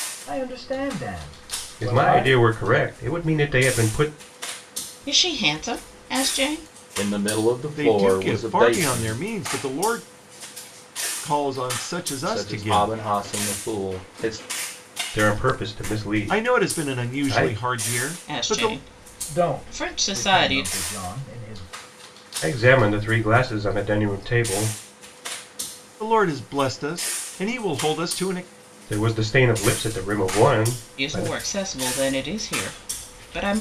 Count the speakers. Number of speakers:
5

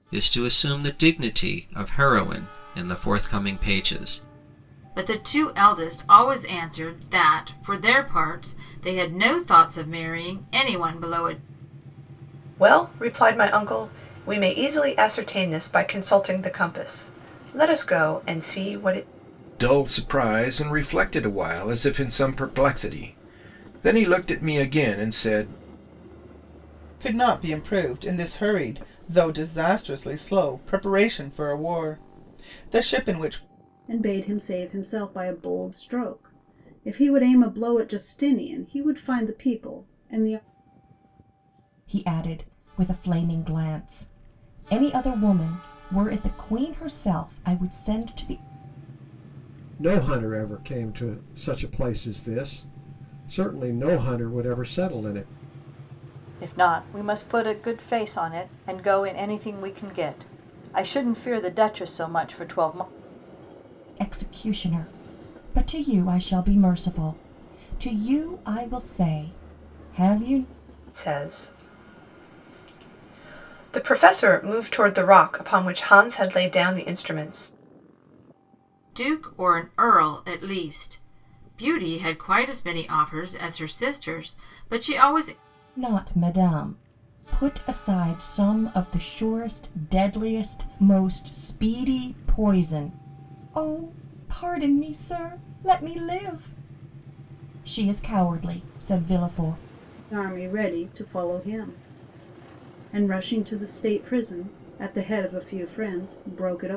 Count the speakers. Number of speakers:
9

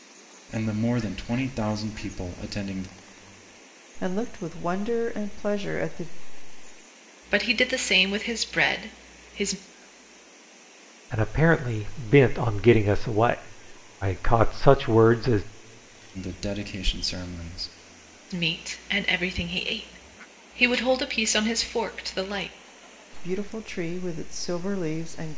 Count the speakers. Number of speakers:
4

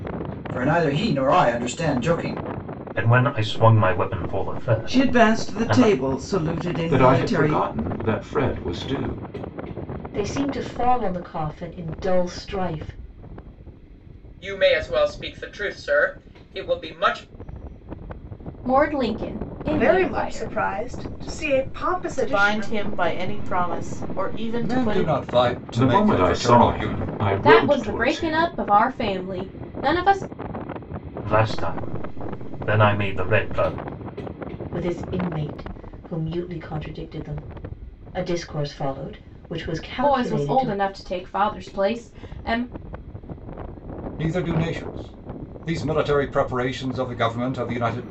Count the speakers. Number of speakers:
10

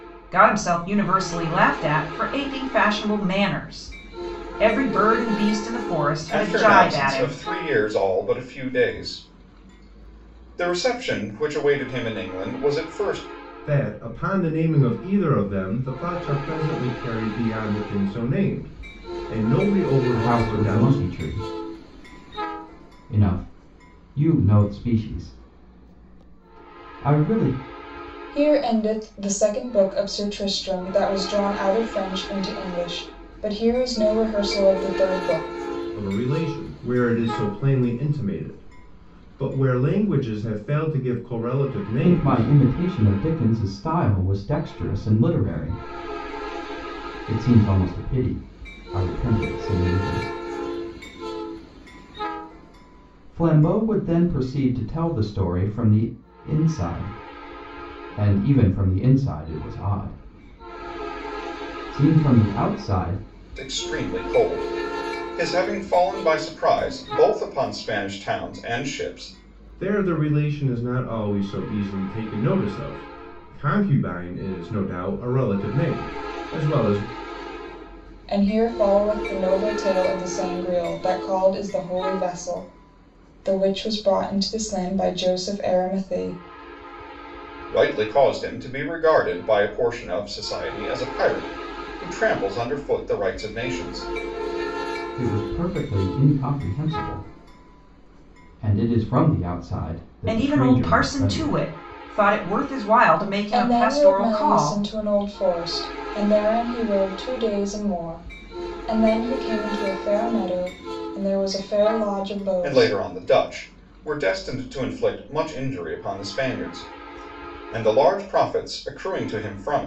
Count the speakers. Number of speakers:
5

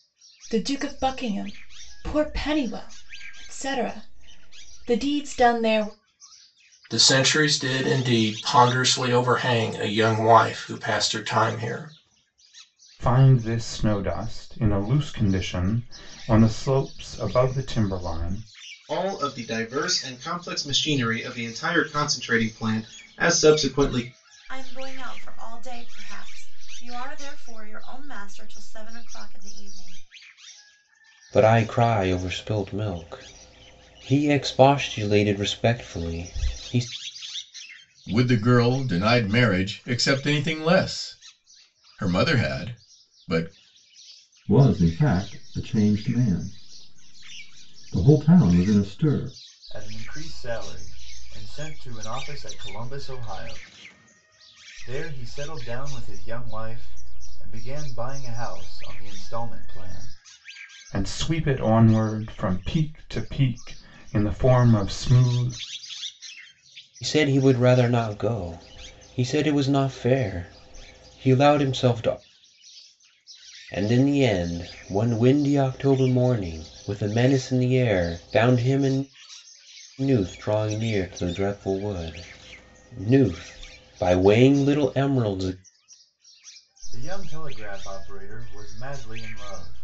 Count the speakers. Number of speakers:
9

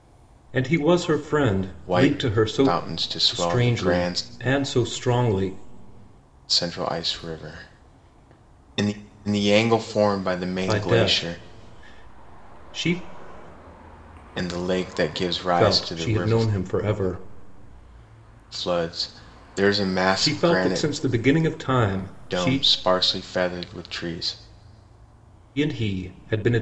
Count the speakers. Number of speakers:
2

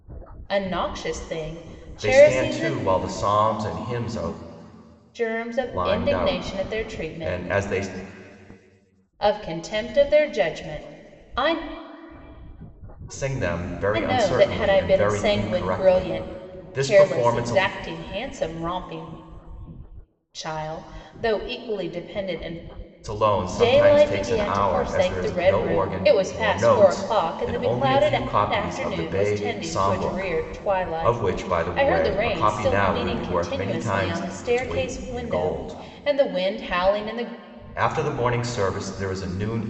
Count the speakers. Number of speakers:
2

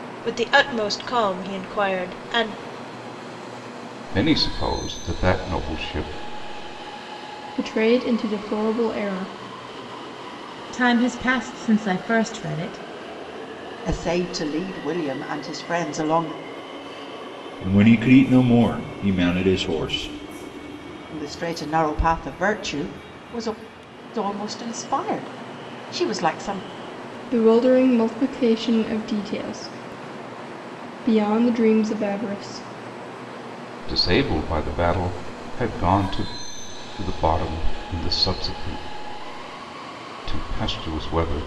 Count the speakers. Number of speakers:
6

